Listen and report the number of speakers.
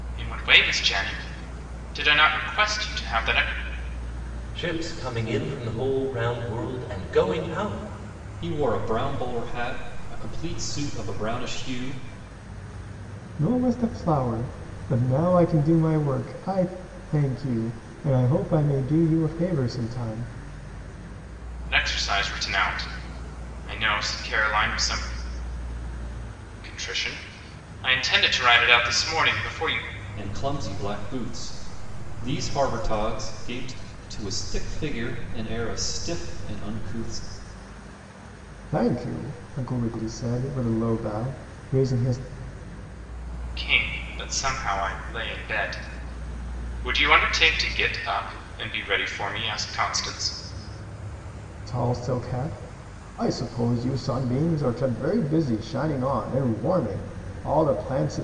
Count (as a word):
four